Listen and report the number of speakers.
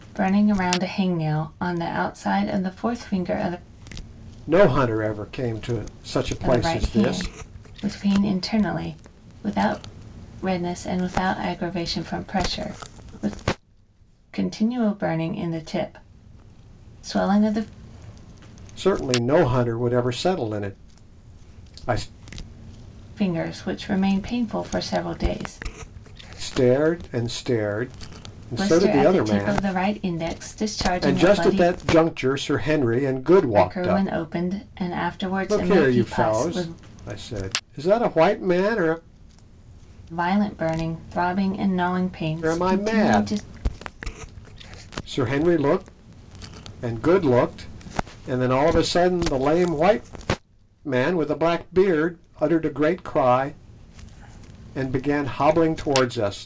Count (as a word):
two